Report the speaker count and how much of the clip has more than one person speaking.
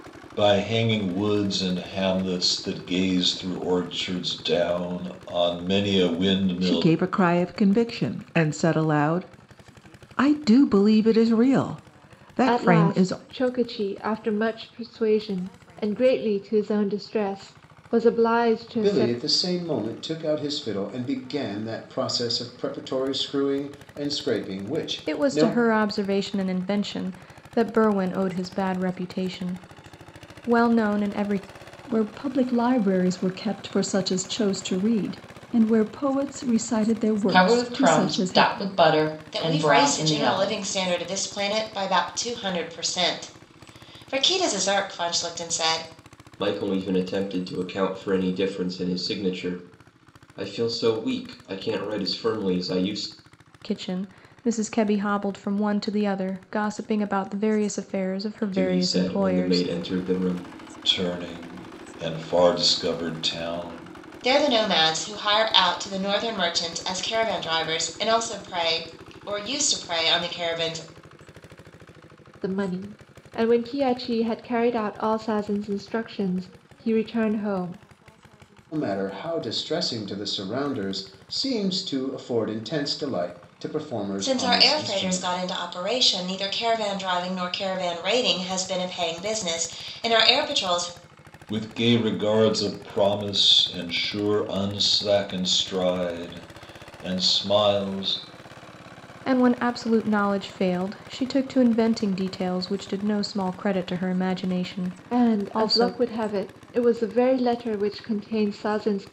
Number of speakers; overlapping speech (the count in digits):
9, about 7%